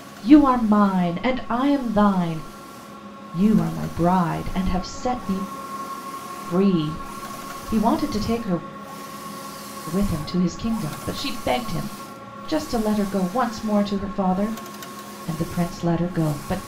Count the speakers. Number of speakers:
1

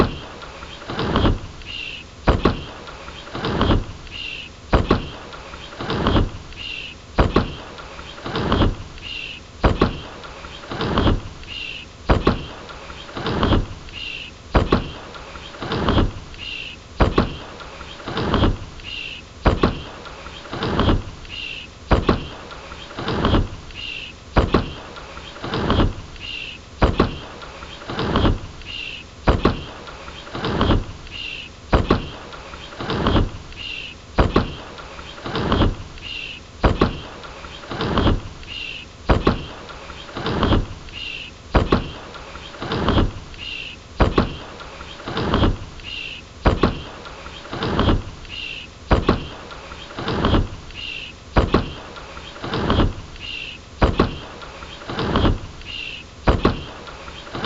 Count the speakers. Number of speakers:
0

